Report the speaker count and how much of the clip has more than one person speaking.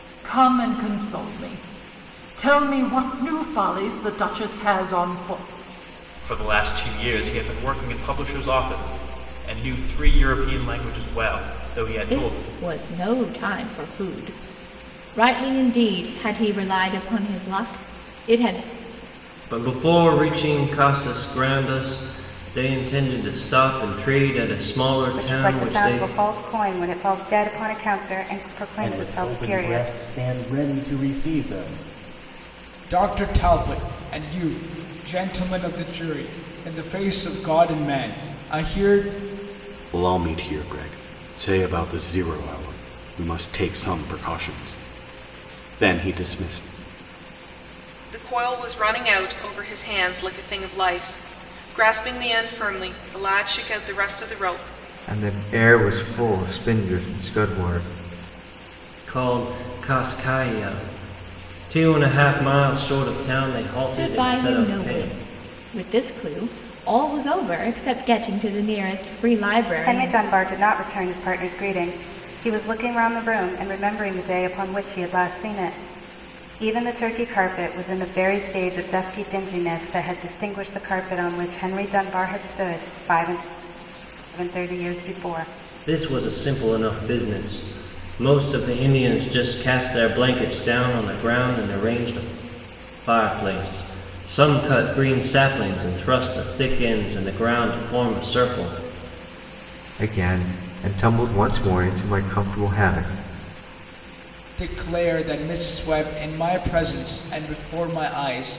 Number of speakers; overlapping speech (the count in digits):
10, about 4%